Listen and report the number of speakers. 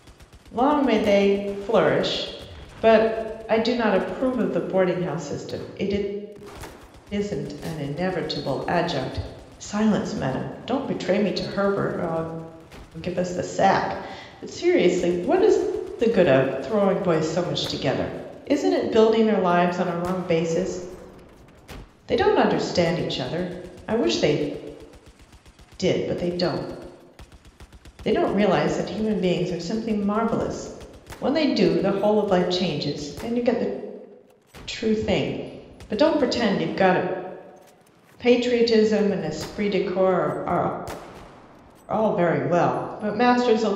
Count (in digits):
1